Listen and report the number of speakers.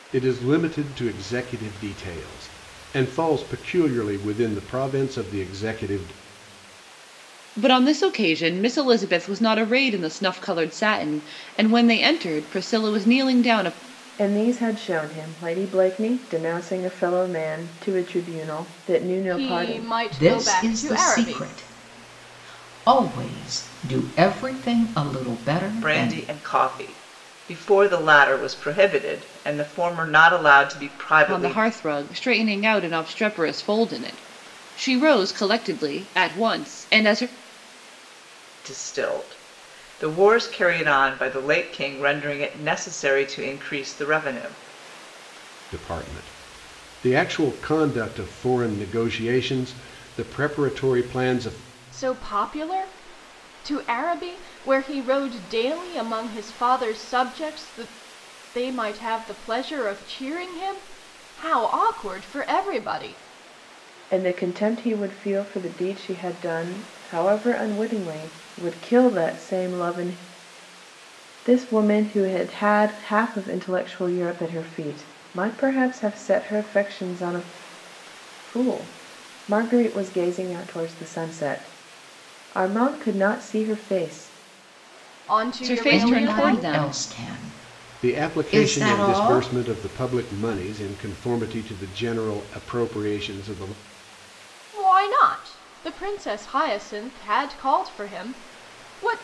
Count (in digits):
6